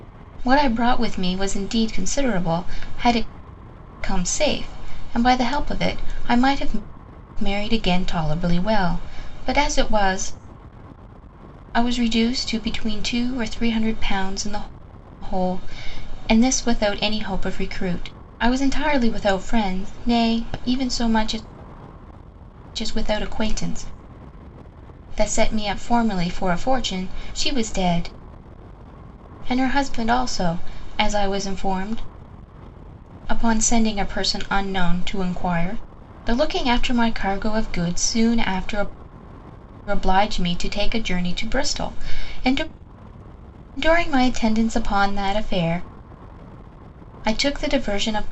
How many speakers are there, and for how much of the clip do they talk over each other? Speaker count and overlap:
one, no overlap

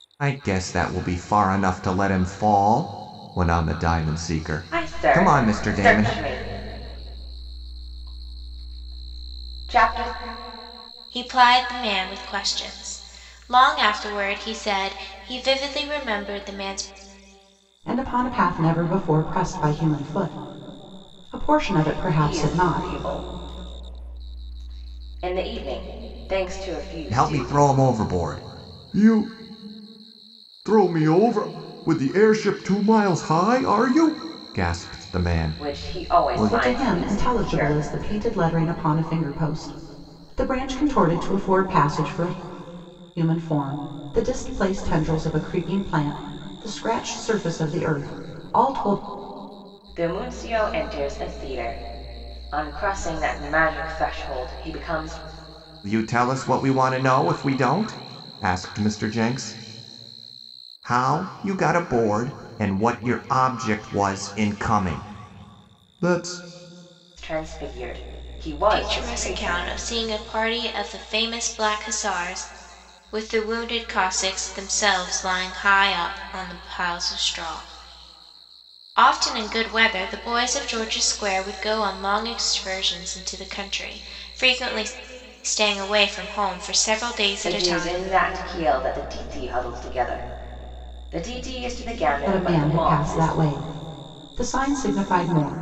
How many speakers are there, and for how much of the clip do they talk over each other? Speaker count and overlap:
four, about 8%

